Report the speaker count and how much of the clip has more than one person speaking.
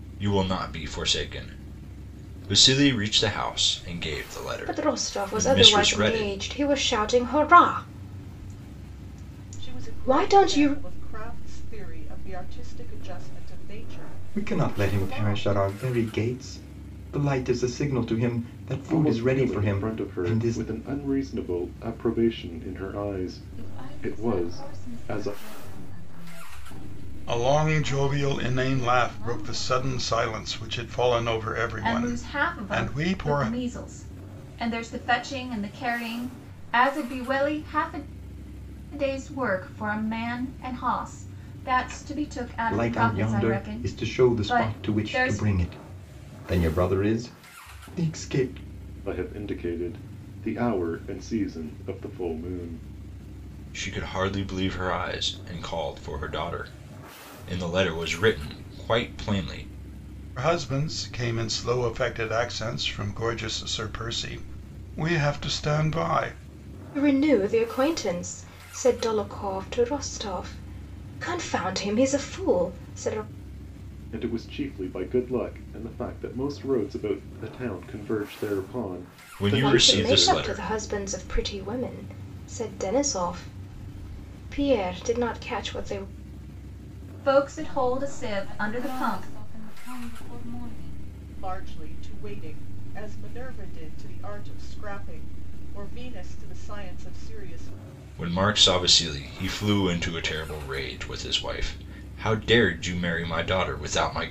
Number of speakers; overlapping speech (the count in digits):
8, about 18%